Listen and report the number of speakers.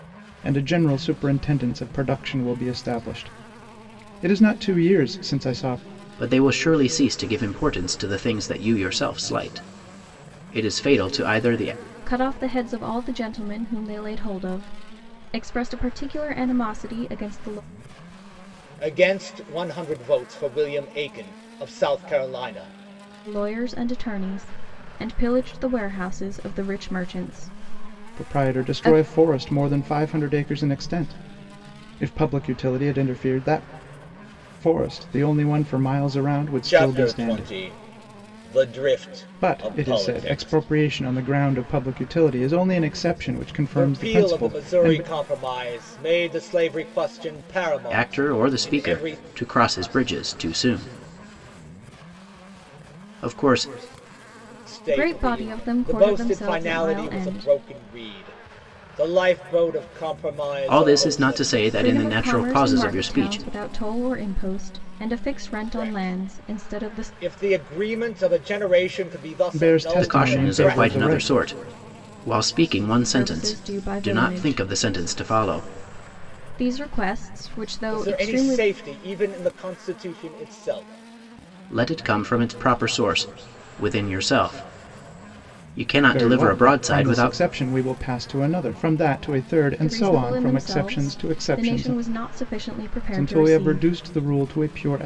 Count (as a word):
four